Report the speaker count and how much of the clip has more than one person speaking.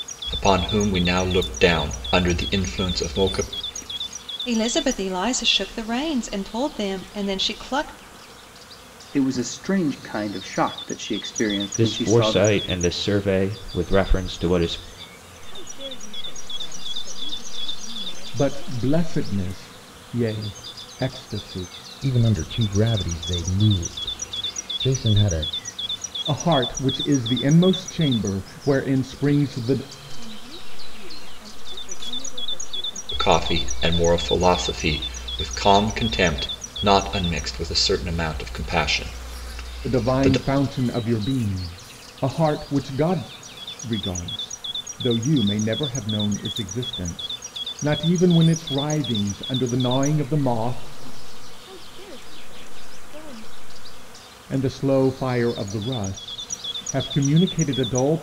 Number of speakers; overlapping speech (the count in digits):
7, about 6%